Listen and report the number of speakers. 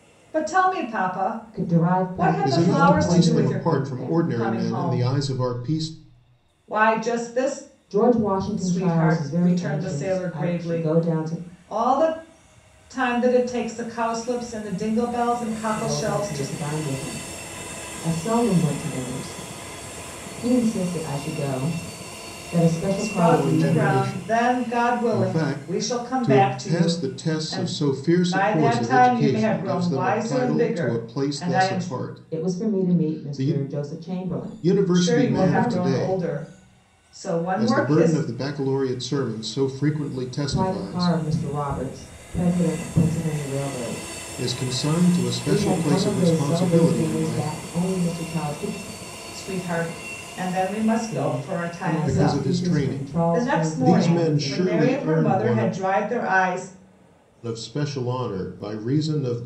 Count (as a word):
three